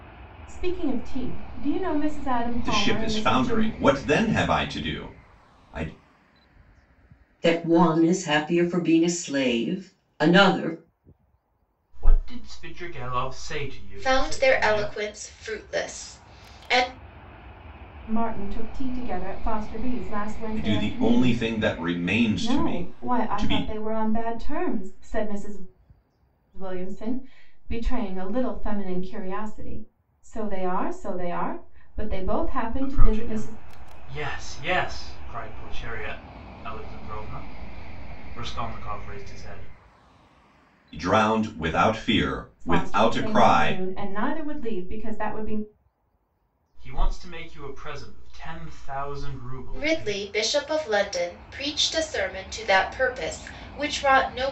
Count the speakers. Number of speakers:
five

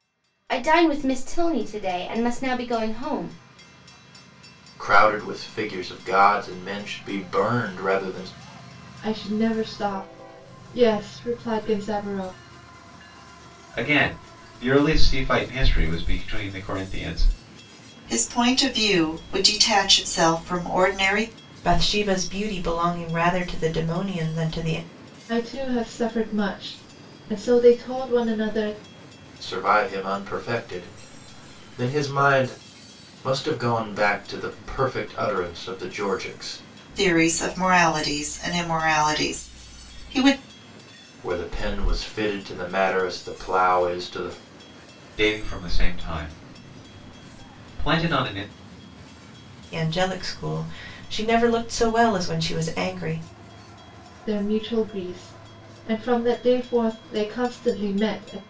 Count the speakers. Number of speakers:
six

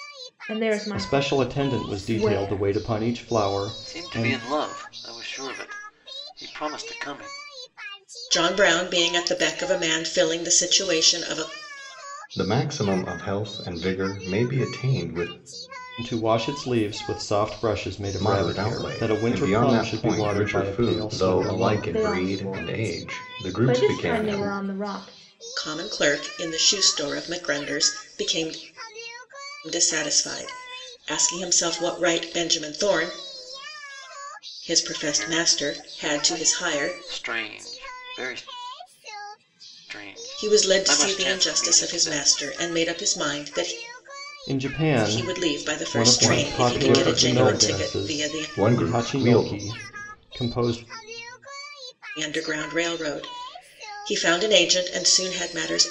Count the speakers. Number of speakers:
five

